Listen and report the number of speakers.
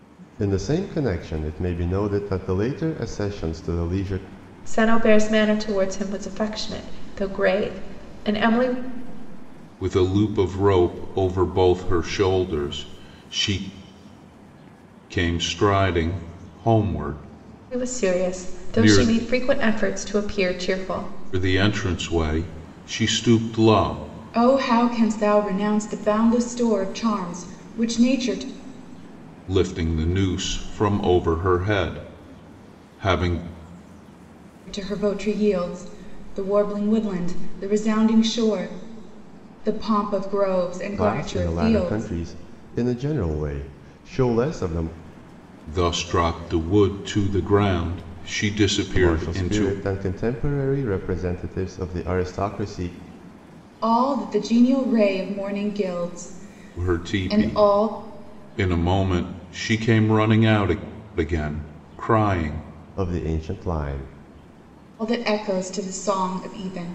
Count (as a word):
three